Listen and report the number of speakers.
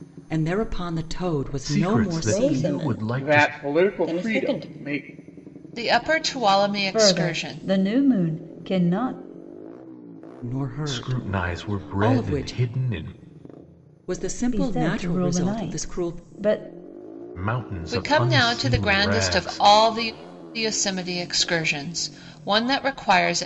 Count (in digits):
6